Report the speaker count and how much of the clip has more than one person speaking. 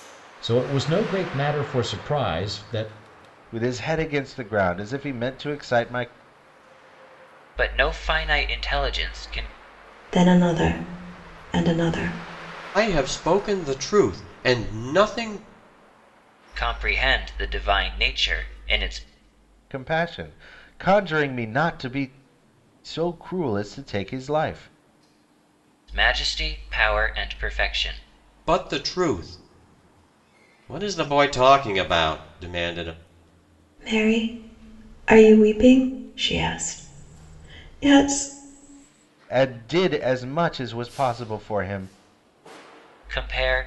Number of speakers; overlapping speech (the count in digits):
5, no overlap